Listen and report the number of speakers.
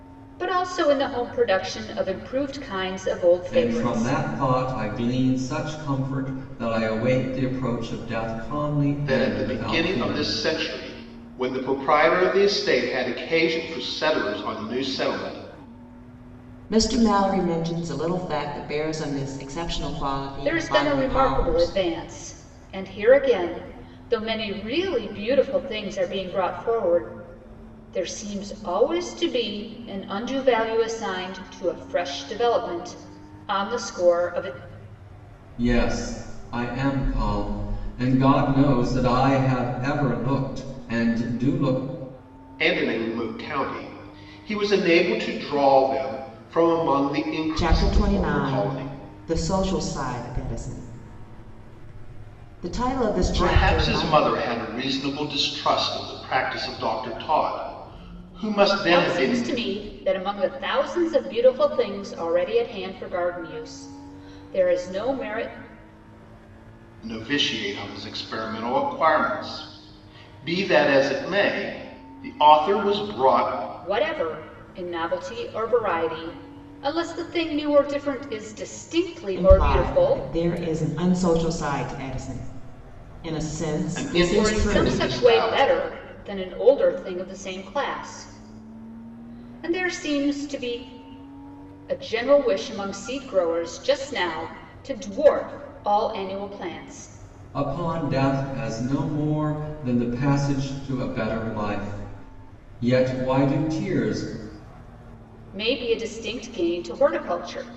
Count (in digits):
4